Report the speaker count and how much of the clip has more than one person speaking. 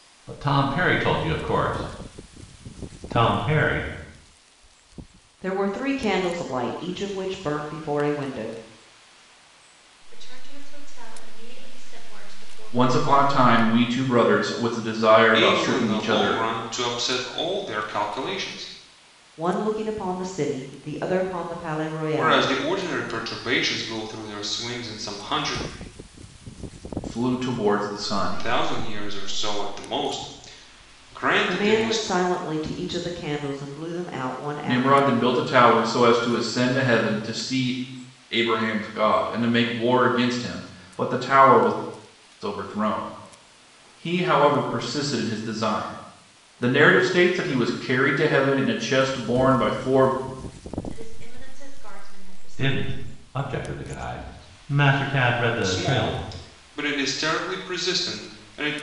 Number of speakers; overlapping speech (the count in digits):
5, about 10%